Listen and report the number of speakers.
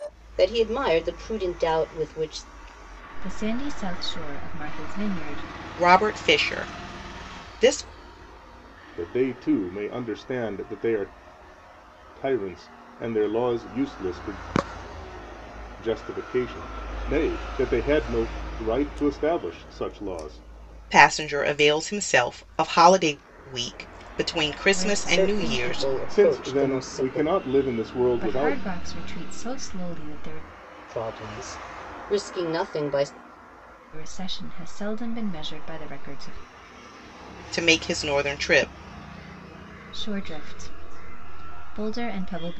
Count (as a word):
four